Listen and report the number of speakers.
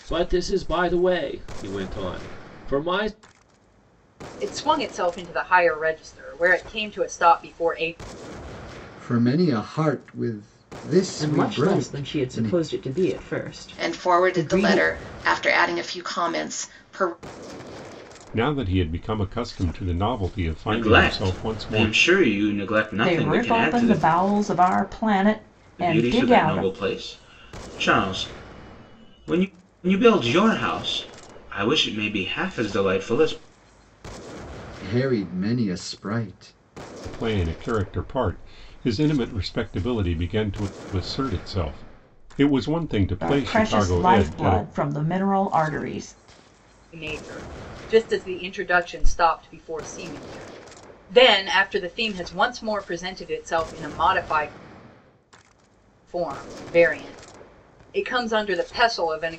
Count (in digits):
8